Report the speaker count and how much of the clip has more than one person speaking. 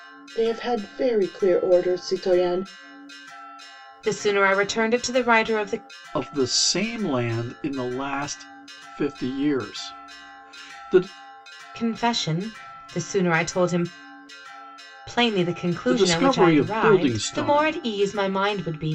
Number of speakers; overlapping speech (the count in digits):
3, about 10%